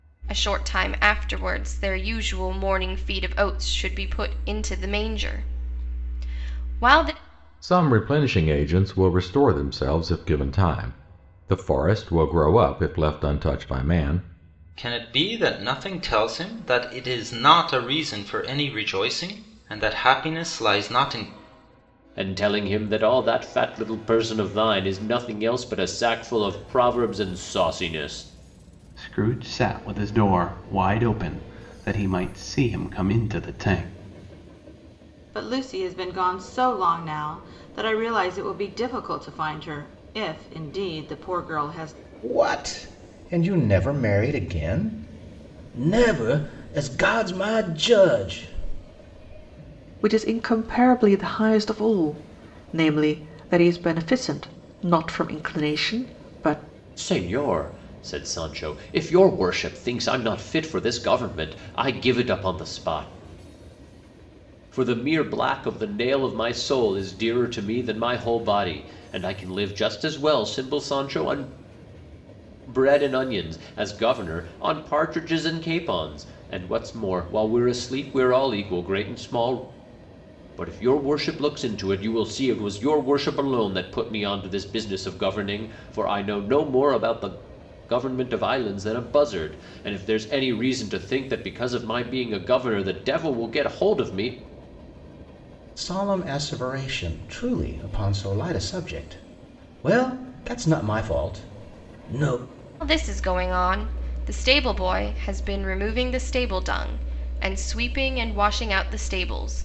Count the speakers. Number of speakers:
8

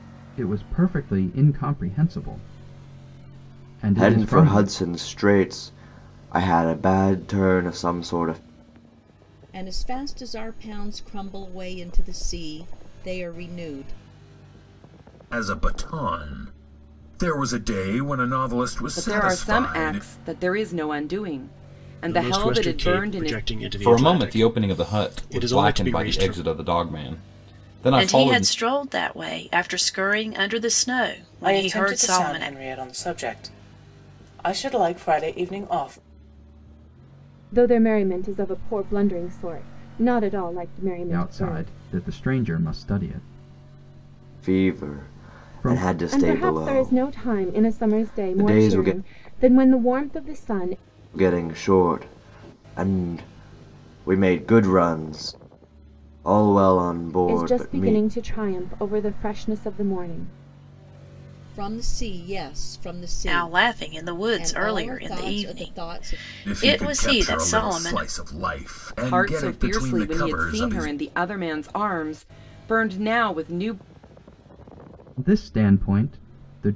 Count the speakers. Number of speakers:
10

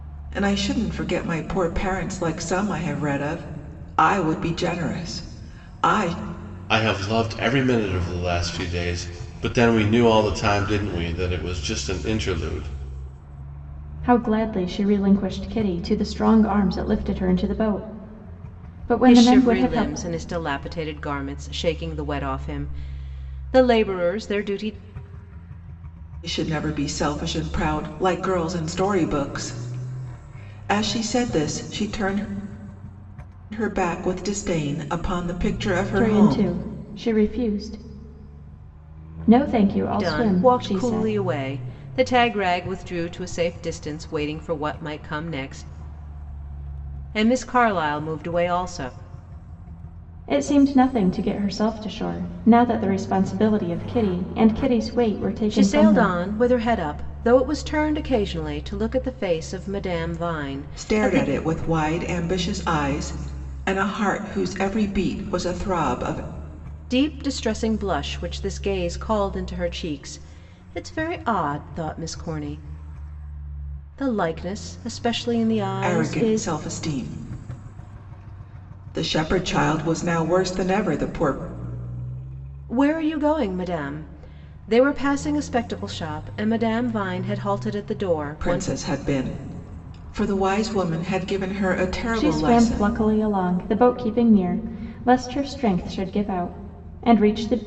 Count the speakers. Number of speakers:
4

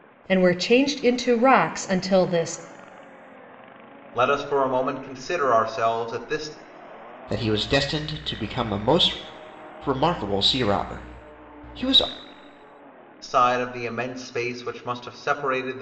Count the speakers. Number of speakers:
3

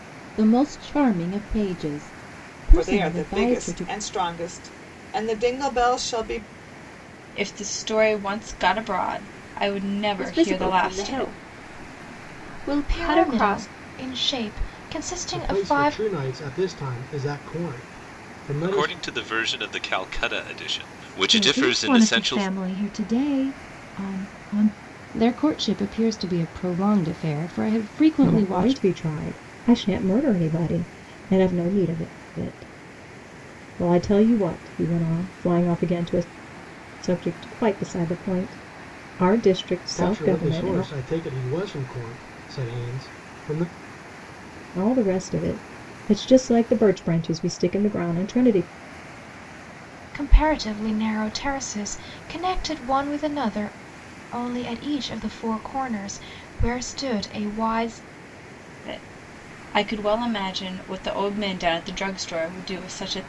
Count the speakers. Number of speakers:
10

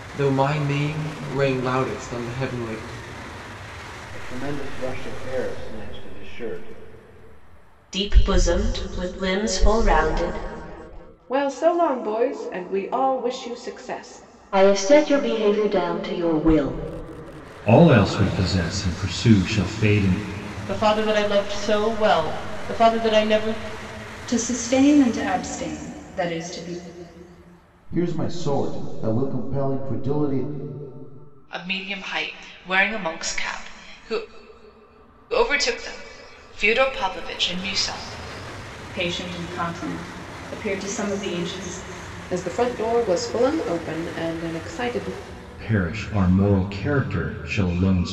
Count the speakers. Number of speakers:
10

